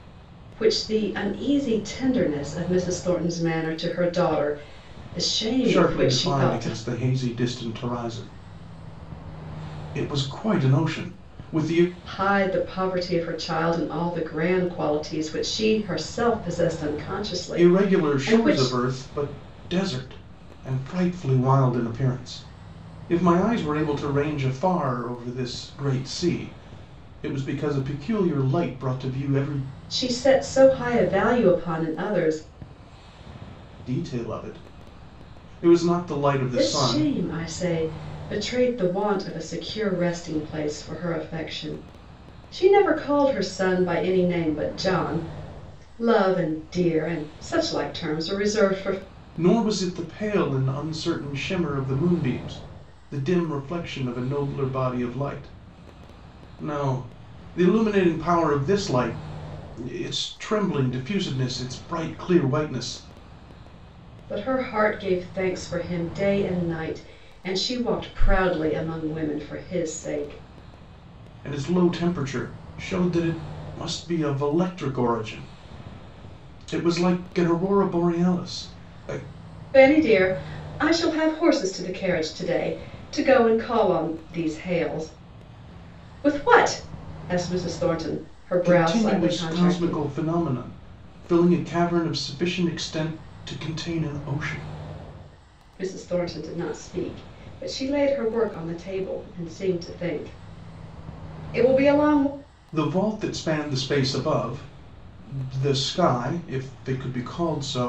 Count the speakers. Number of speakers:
2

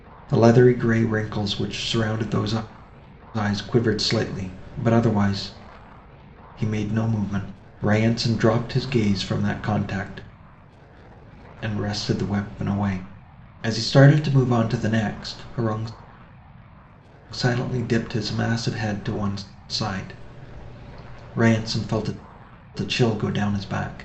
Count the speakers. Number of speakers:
1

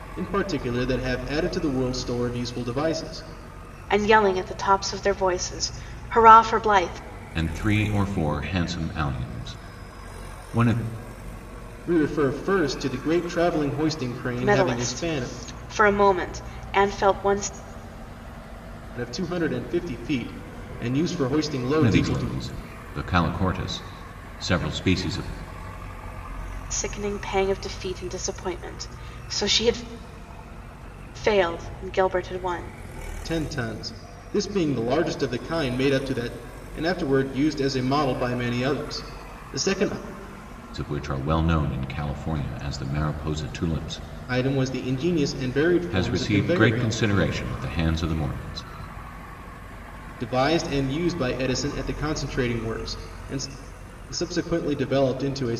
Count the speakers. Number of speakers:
3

